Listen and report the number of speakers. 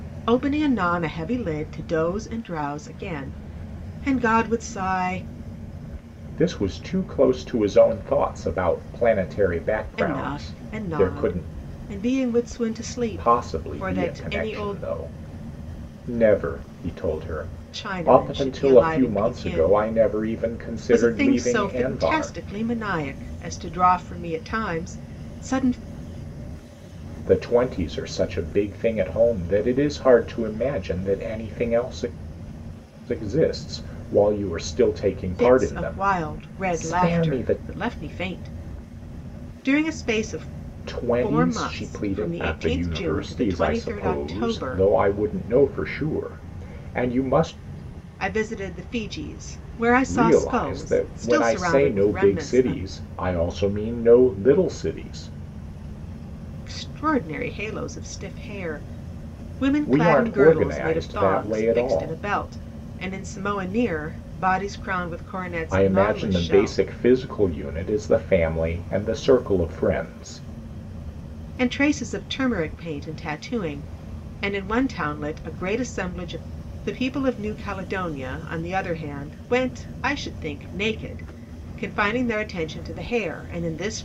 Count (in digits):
2